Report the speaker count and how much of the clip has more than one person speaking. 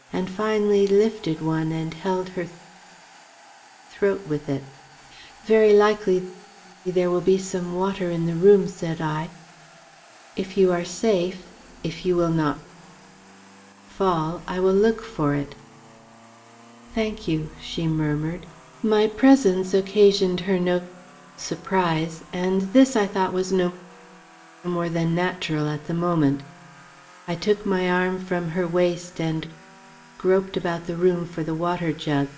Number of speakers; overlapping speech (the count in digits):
1, no overlap